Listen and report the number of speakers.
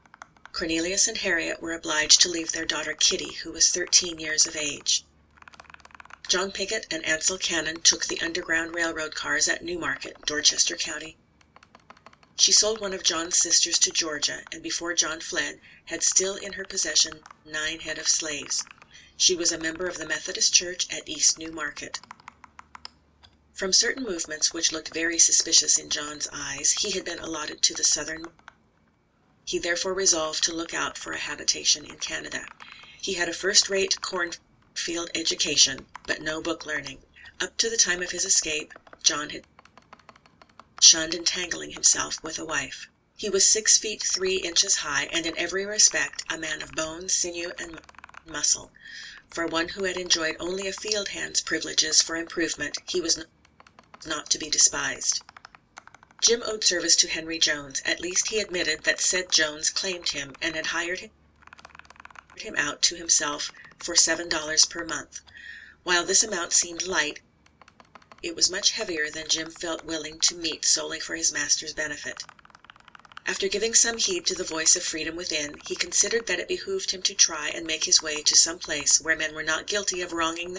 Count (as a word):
one